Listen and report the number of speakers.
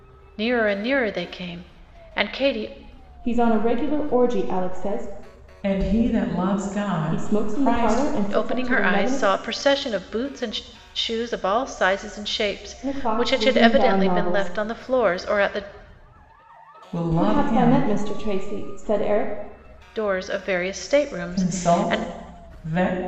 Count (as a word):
three